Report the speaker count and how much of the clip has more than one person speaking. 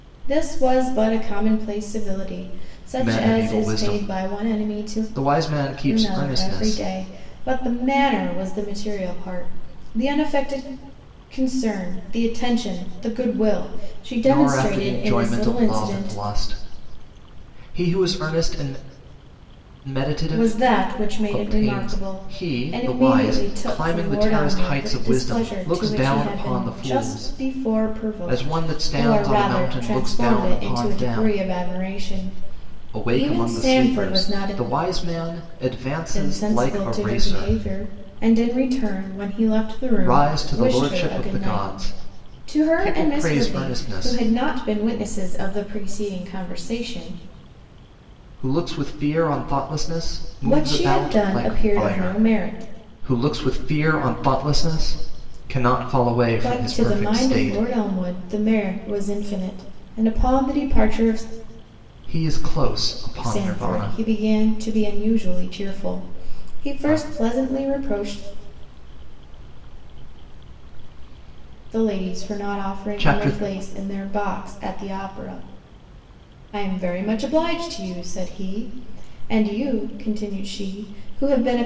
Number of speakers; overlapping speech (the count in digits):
2, about 35%